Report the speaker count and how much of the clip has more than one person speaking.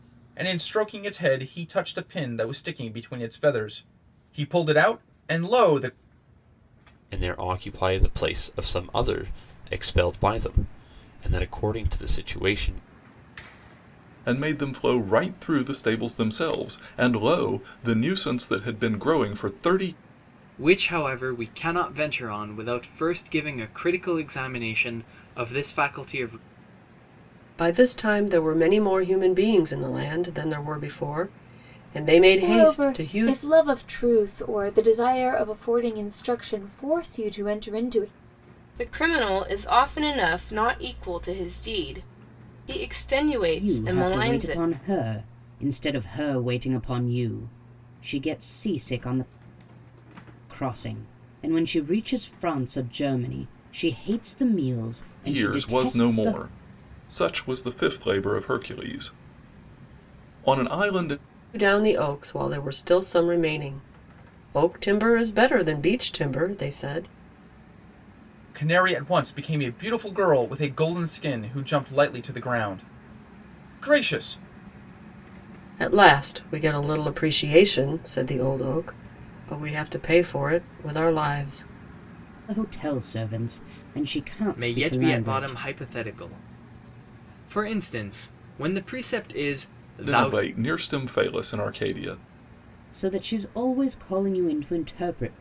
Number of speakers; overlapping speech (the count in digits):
8, about 5%